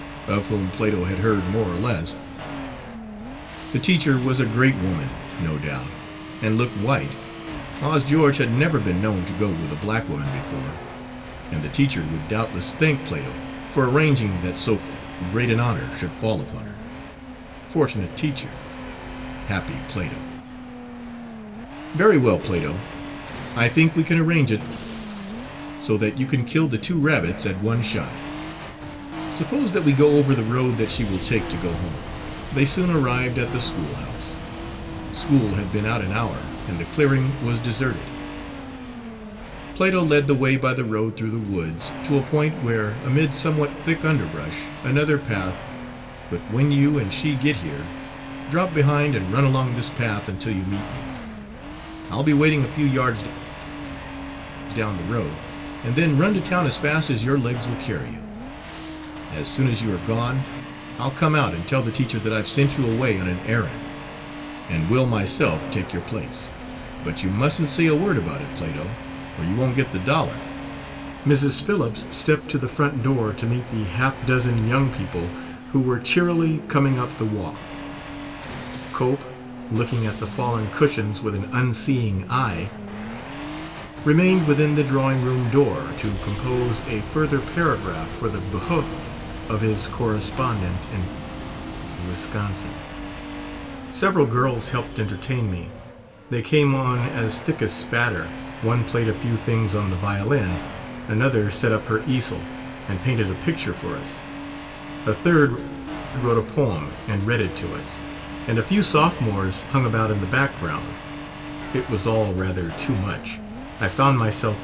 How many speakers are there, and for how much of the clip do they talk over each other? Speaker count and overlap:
1, no overlap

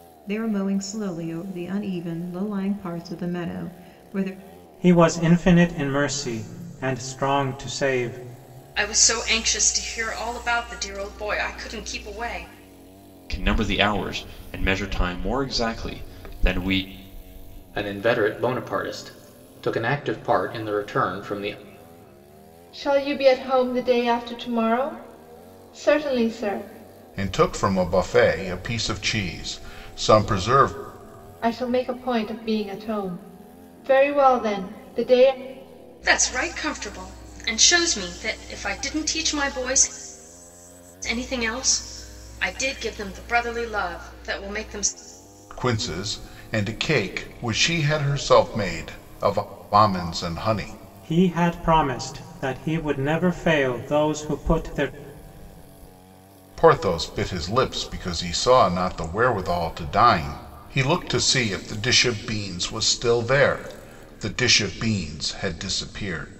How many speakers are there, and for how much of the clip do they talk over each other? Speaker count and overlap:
7, no overlap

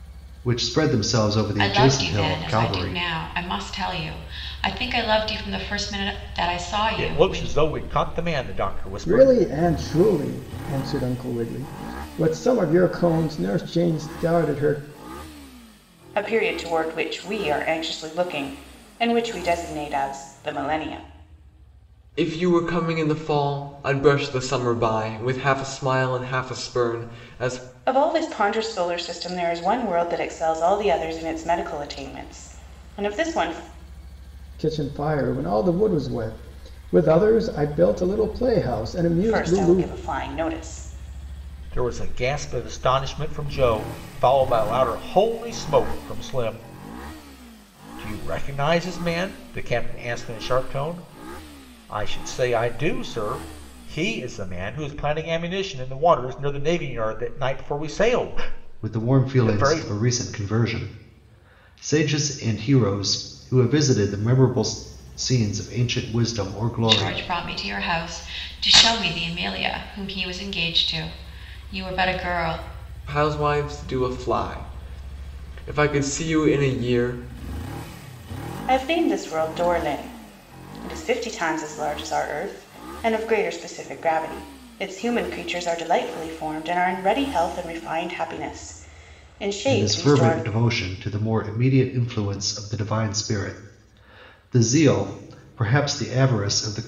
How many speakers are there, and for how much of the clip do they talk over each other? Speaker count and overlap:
6, about 5%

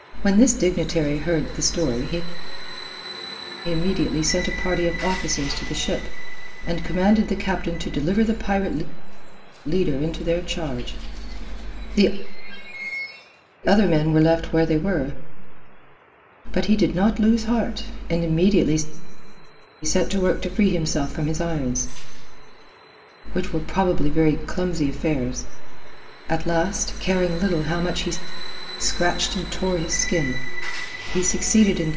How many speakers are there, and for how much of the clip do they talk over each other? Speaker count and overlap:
1, no overlap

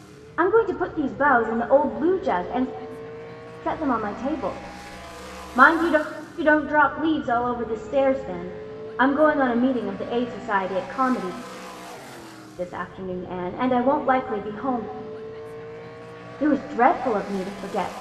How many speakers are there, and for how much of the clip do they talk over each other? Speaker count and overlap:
1, no overlap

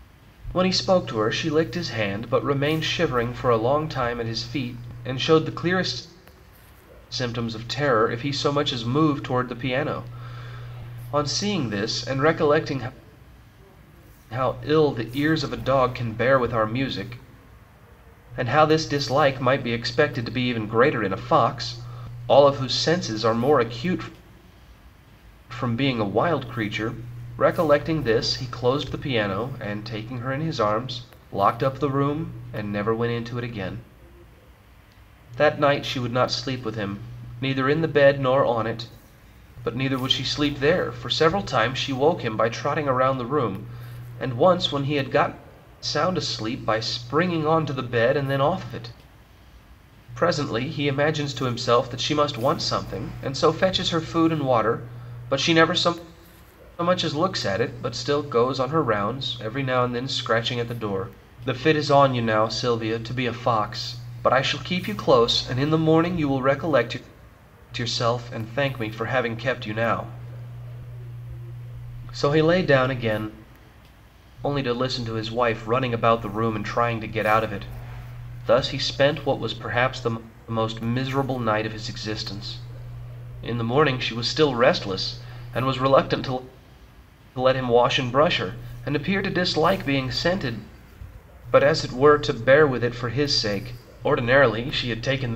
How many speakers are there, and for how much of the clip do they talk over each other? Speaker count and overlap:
1, no overlap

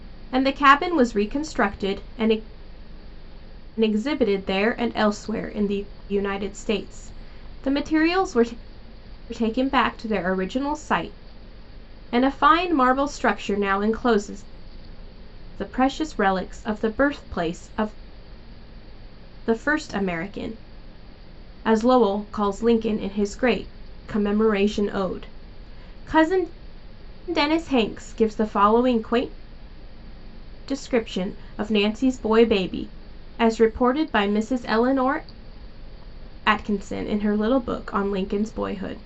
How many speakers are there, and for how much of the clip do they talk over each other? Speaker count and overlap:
1, no overlap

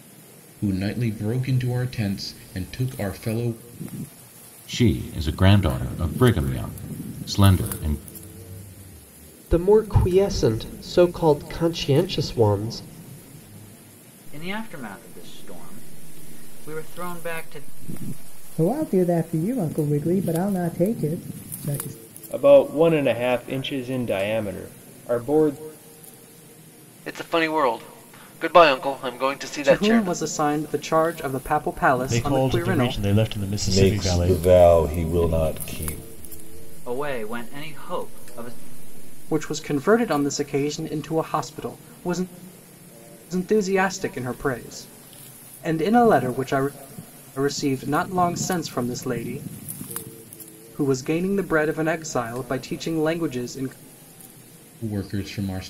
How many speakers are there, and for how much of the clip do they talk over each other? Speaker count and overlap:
10, about 6%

